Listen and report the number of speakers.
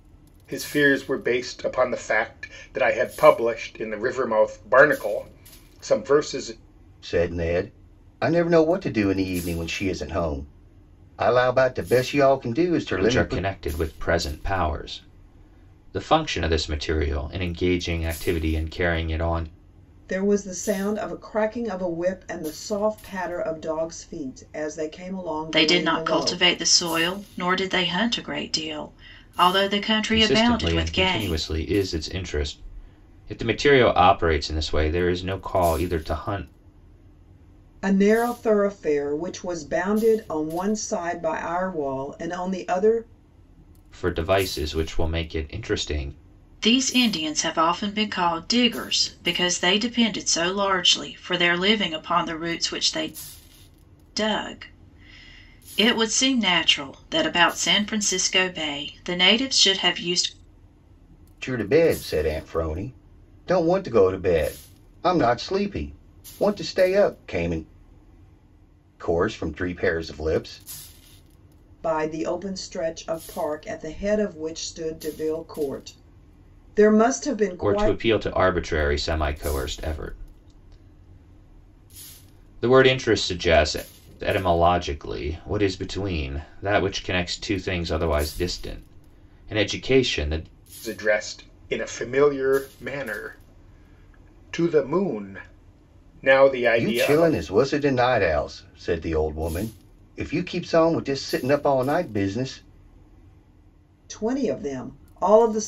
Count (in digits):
5